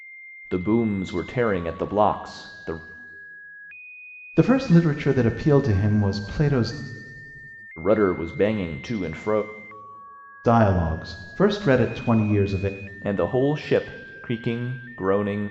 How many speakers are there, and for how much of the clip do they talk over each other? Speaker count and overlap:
2, no overlap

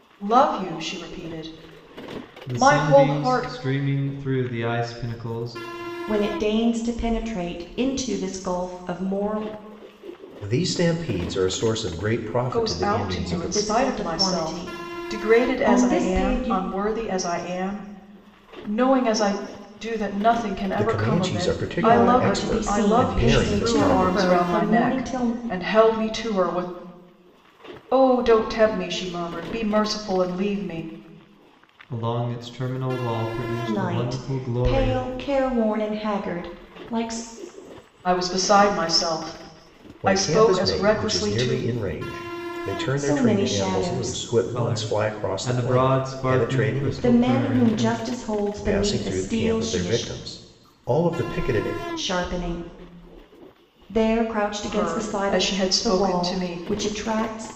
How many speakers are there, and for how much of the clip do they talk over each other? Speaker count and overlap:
4, about 36%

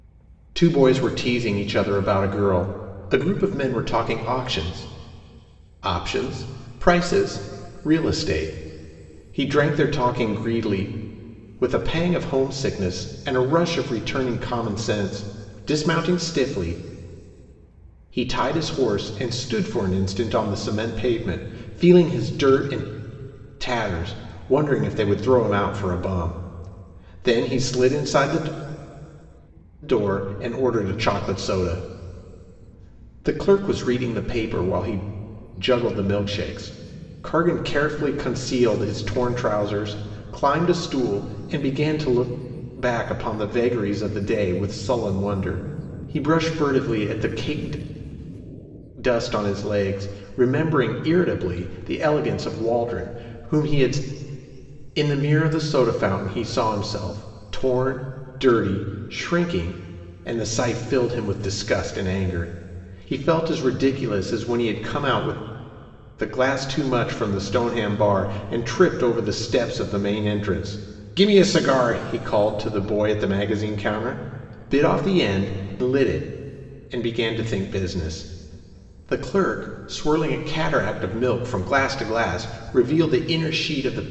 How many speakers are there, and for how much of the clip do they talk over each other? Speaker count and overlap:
1, no overlap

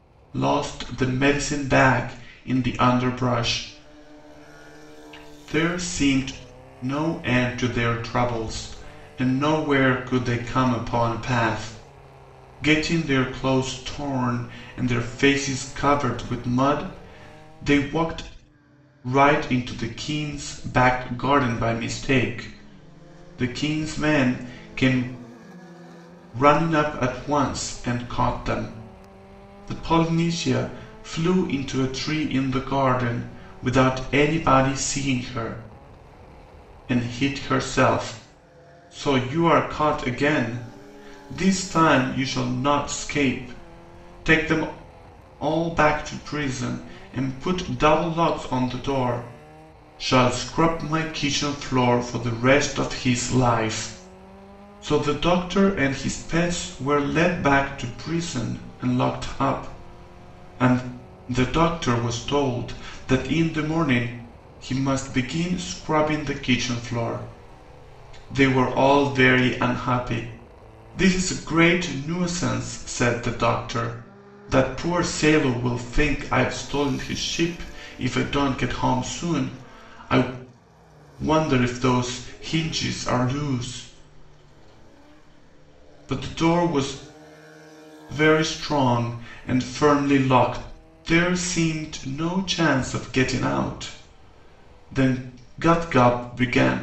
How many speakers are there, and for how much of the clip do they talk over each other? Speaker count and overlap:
1, no overlap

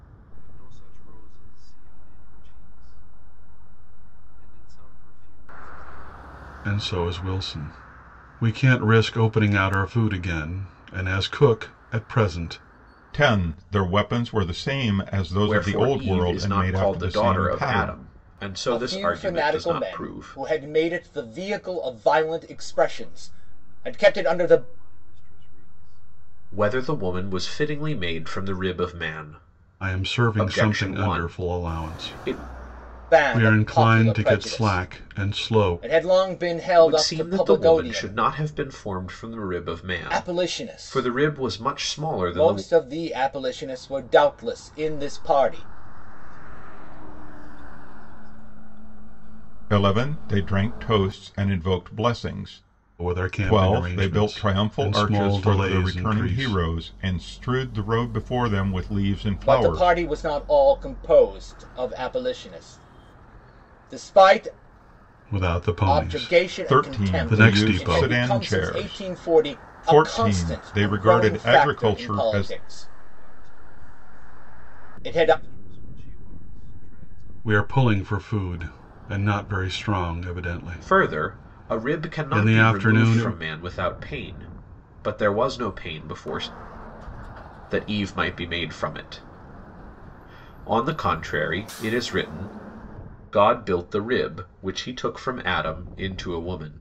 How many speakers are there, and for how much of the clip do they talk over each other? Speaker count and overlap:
5, about 38%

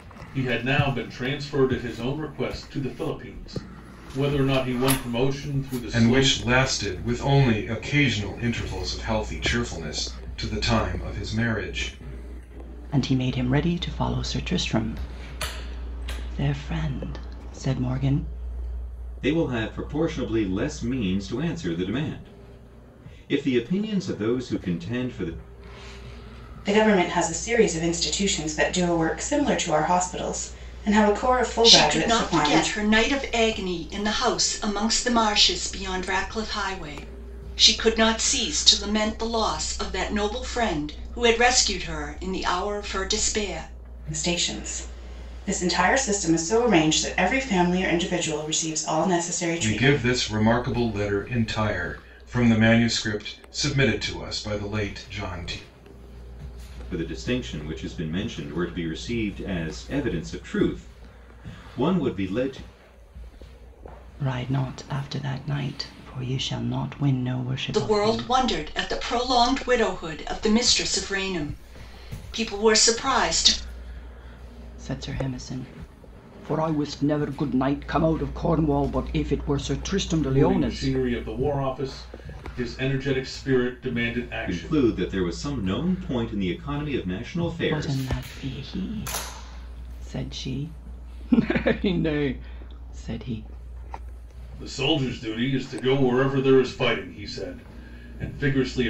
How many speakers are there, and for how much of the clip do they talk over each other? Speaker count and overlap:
6, about 4%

